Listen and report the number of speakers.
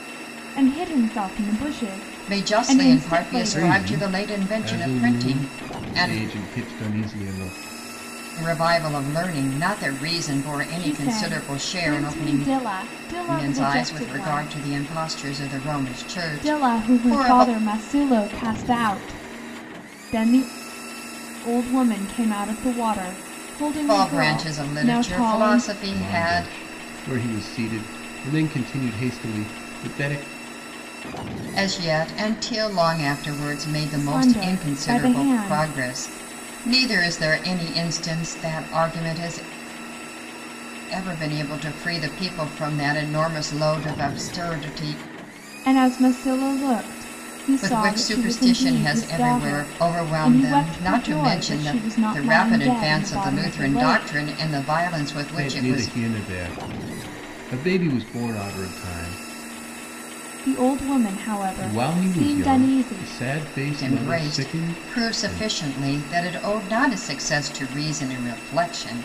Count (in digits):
3